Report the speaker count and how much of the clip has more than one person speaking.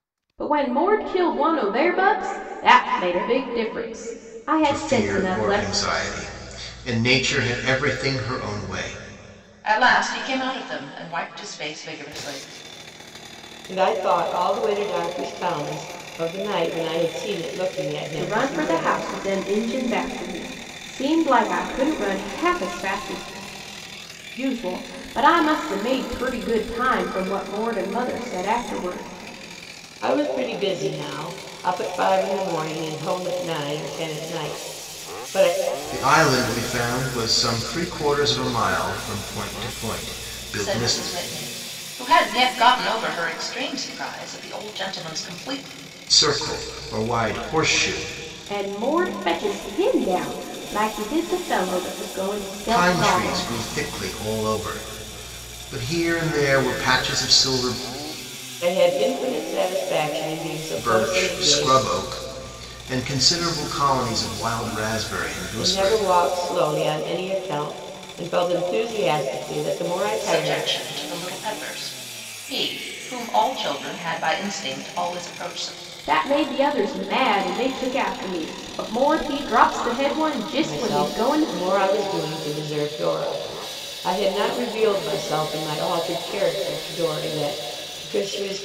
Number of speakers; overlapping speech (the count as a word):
four, about 7%